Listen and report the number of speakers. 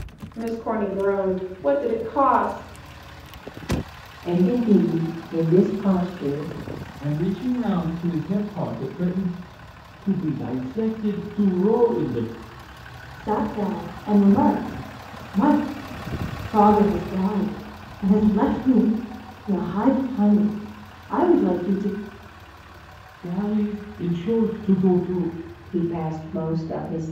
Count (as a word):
five